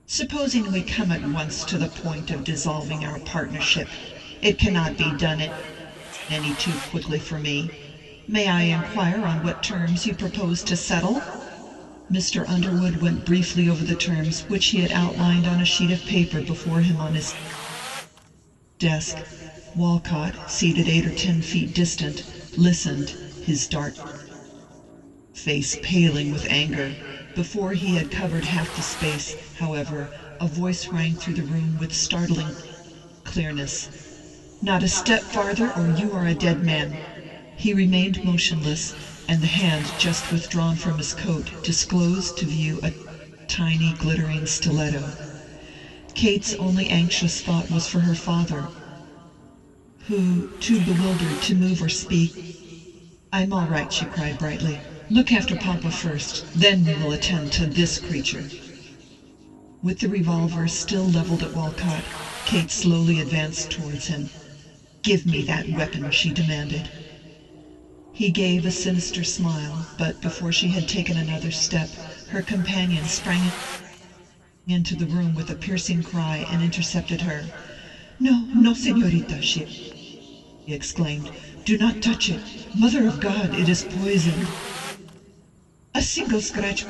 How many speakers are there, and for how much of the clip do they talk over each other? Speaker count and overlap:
one, no overlap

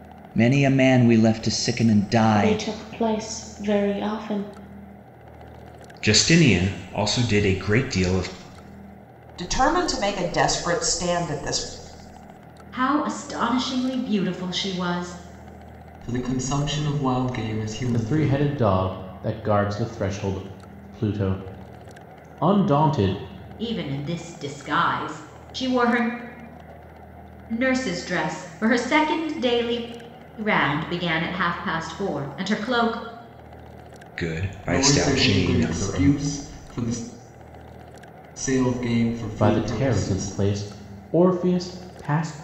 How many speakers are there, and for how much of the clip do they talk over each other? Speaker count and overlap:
seven, about 8%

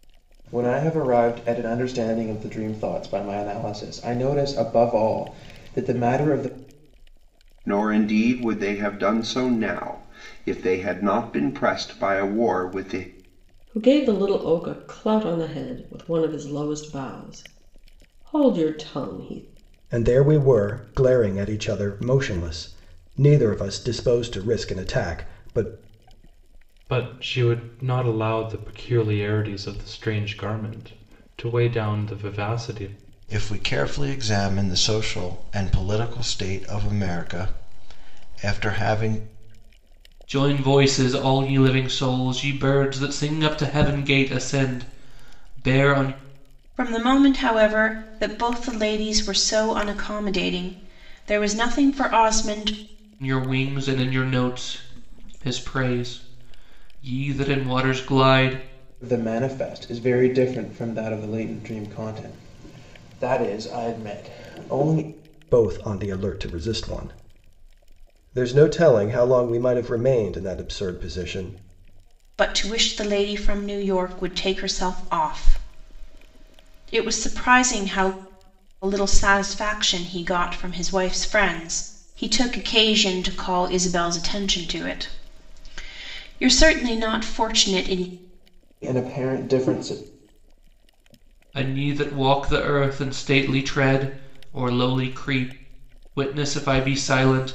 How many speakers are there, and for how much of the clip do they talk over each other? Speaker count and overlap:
eight, no overlap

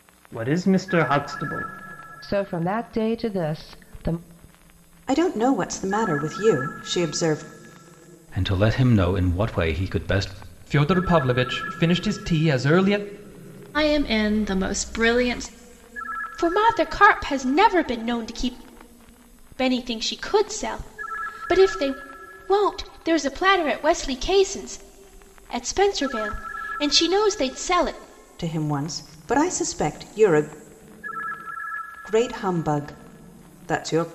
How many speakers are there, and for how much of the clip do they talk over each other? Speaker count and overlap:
seven, no overlap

